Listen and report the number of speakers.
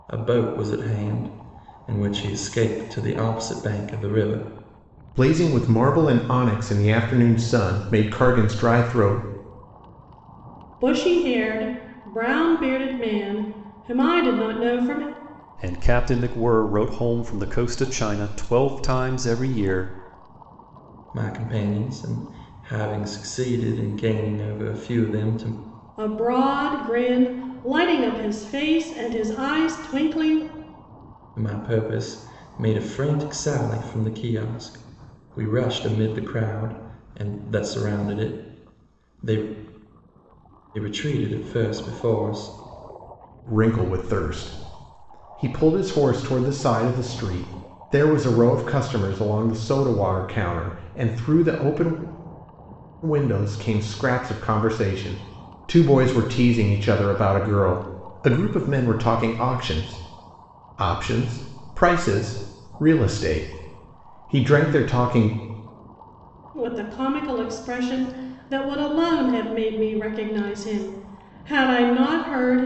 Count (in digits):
4